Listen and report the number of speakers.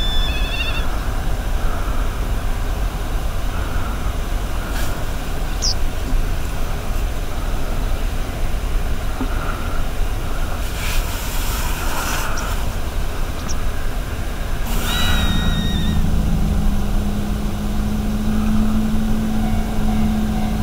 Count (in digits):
0